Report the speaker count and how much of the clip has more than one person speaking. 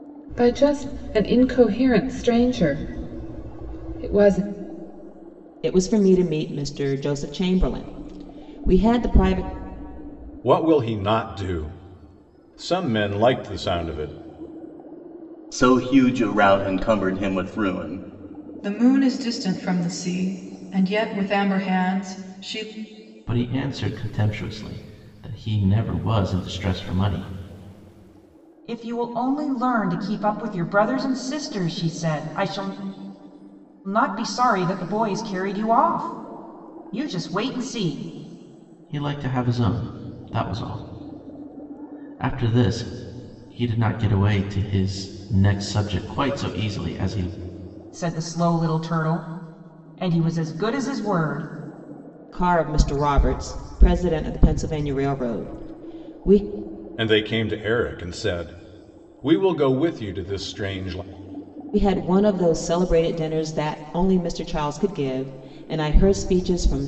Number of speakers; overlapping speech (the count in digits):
7, no overlap